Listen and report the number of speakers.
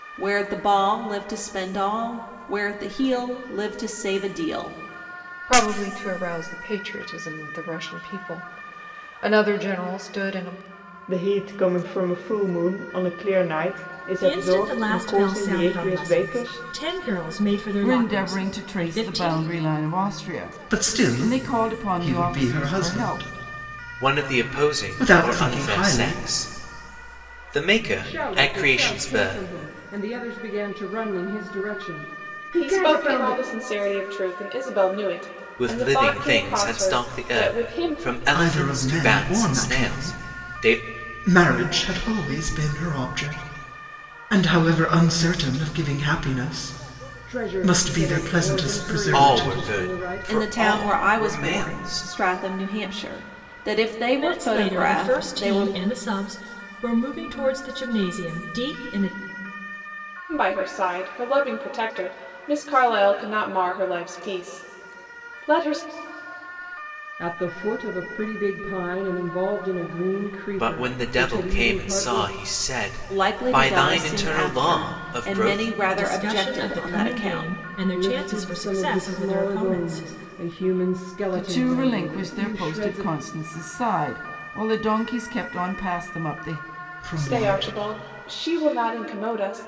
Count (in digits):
9